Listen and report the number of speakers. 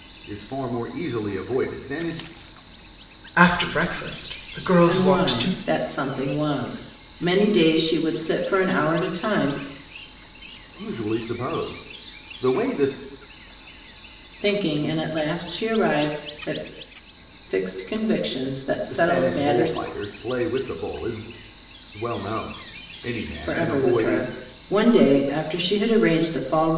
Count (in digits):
3